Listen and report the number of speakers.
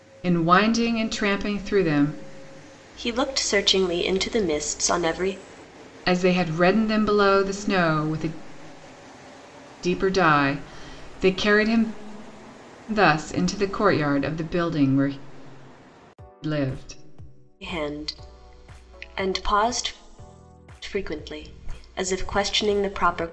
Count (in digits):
2